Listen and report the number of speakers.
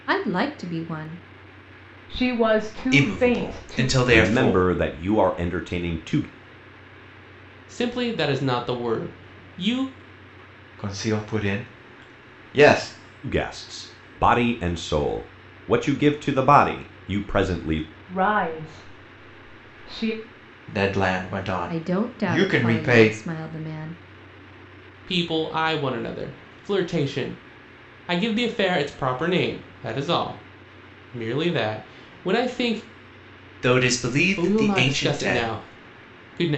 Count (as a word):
six